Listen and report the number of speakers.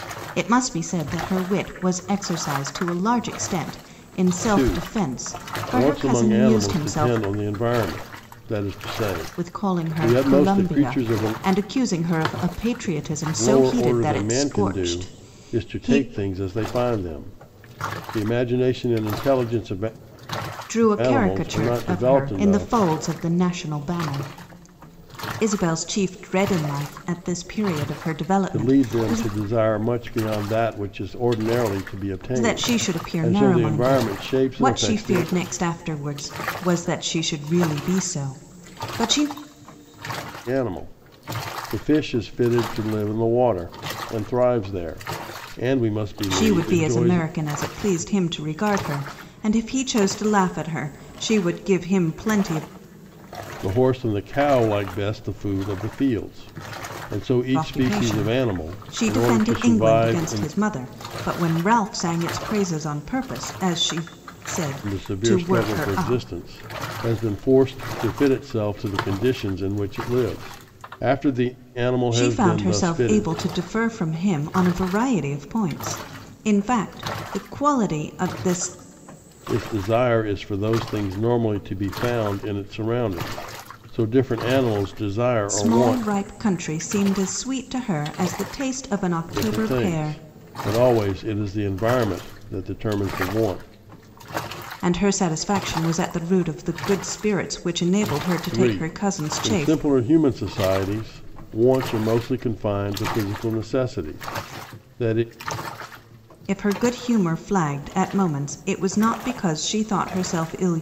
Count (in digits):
2